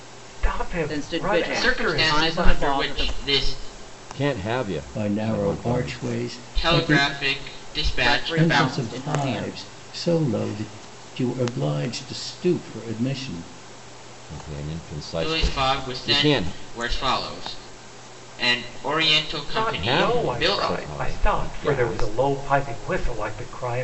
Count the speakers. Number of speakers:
5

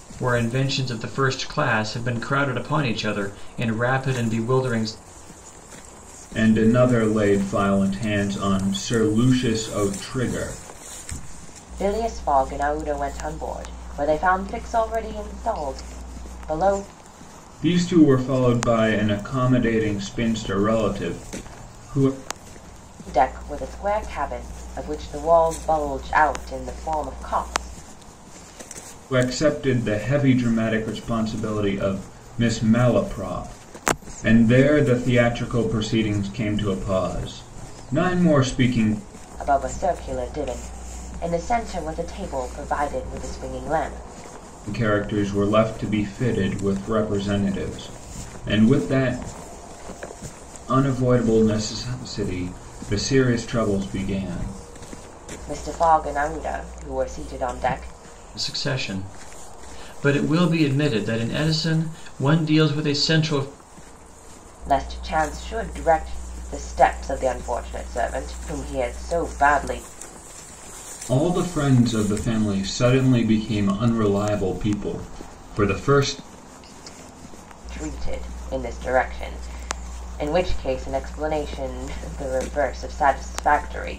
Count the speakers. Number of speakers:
3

